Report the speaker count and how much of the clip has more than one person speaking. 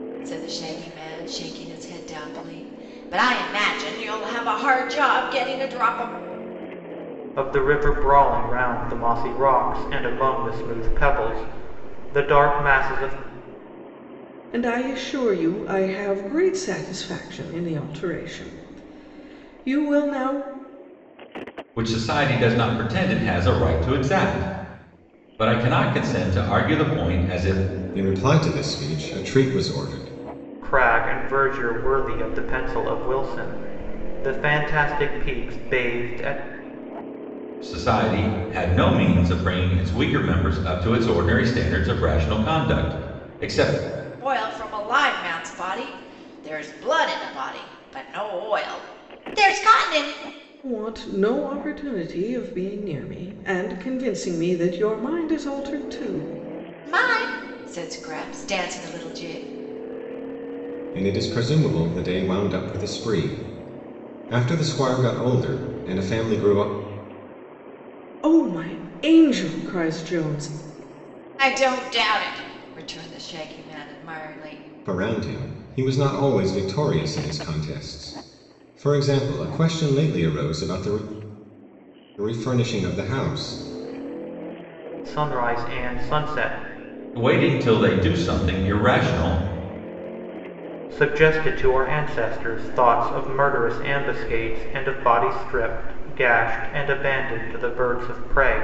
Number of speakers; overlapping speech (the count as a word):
five, no overlap